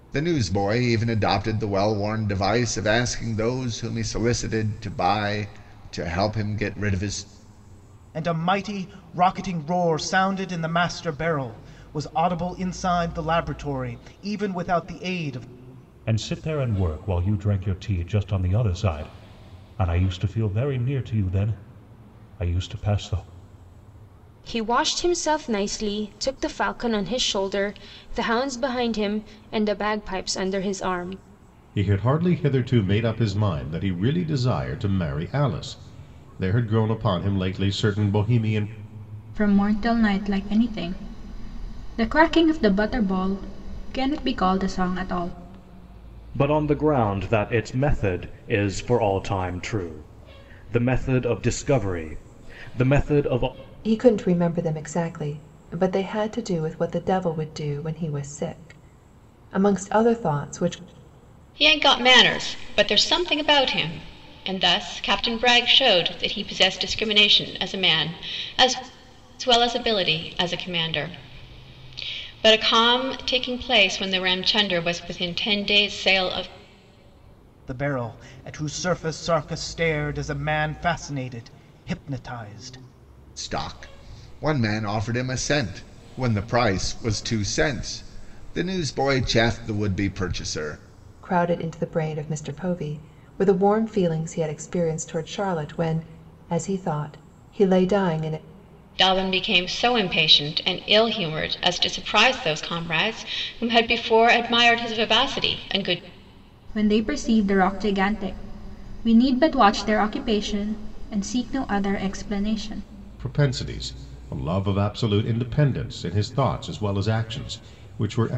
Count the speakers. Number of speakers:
9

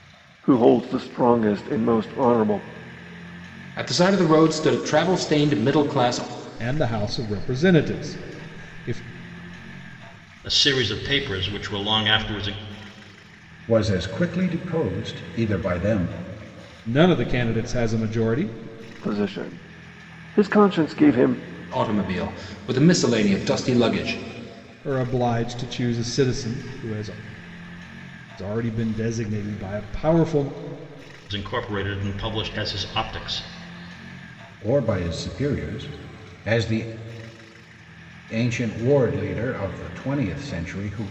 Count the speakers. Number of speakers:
5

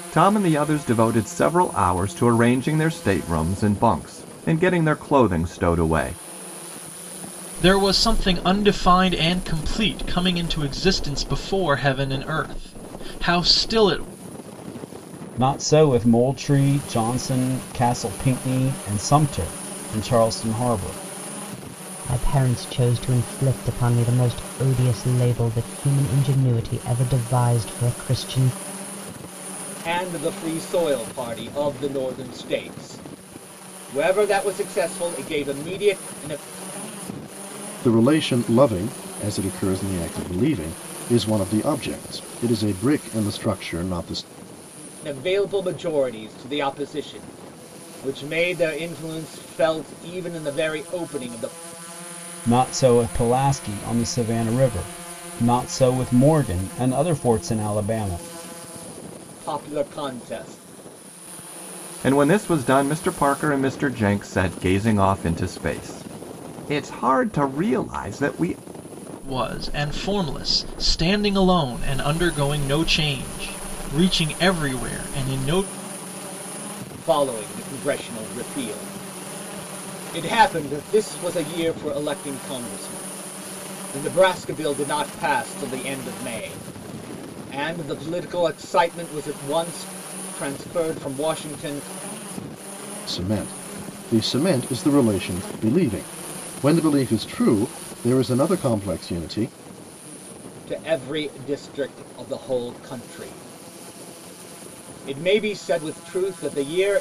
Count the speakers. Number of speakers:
6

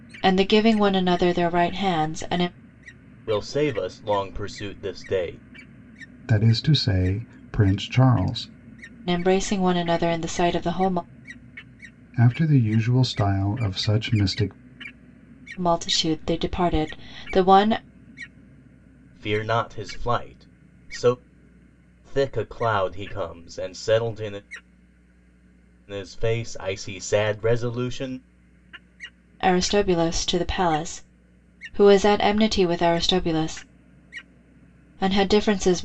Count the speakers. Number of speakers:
3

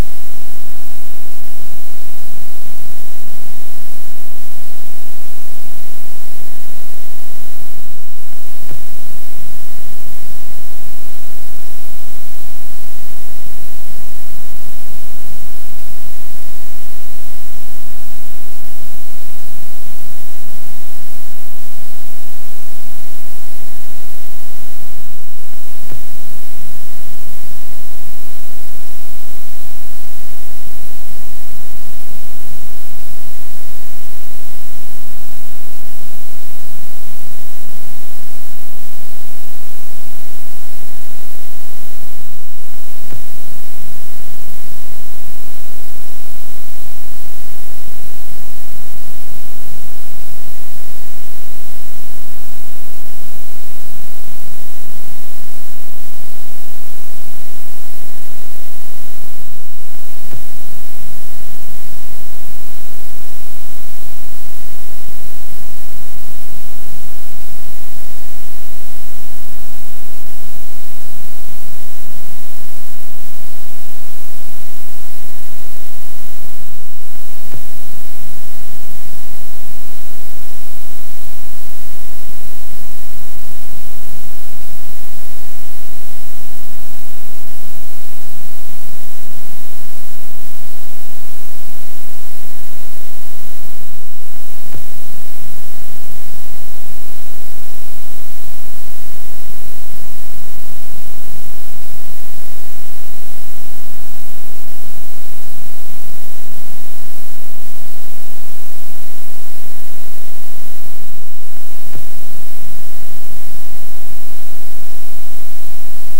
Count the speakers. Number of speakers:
0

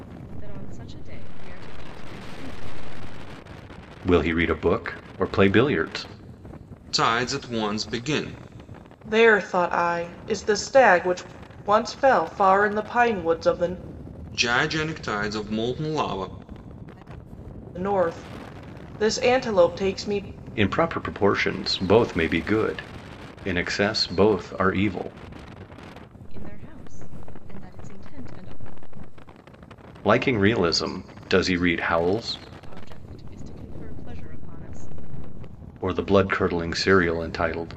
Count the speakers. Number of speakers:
4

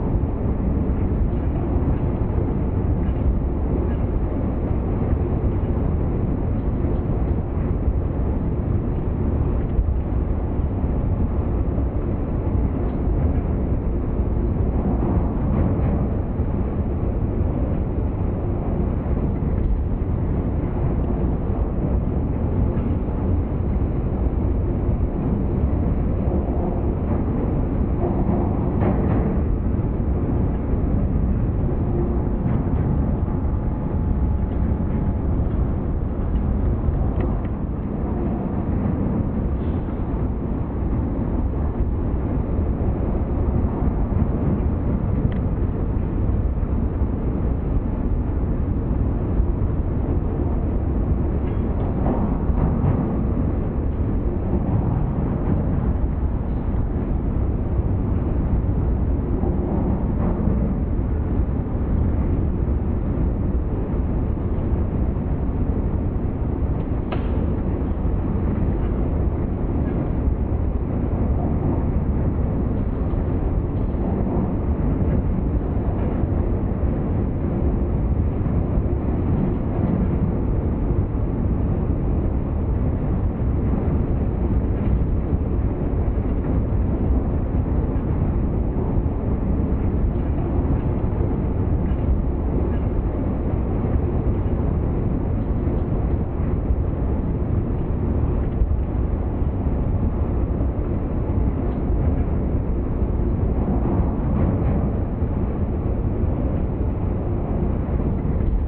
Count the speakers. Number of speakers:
0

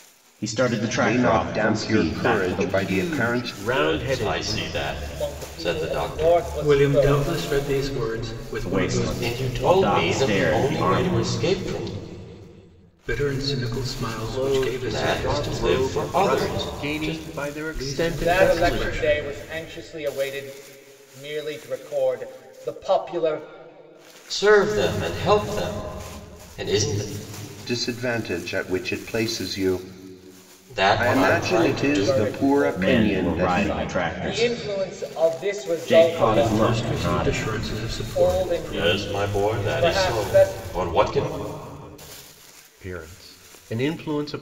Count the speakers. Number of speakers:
6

